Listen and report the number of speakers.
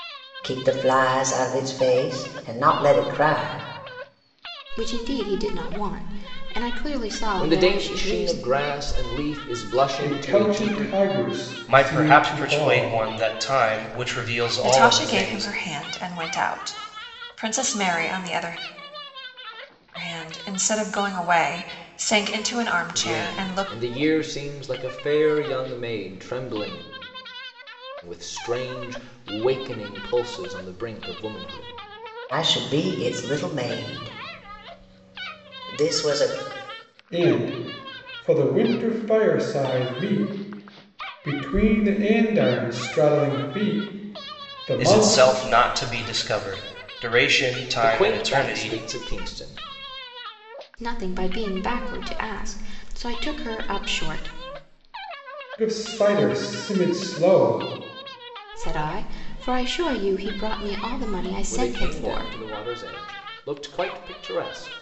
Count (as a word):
six